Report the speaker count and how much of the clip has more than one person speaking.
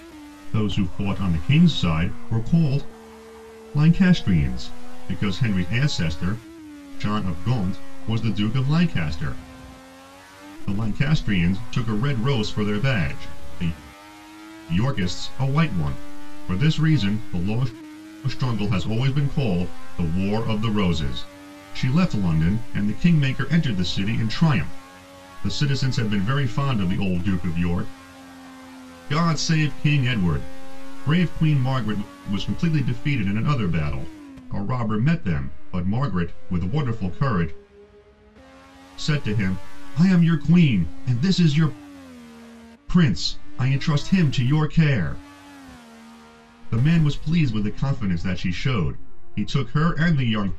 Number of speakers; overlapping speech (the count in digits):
1, no overlap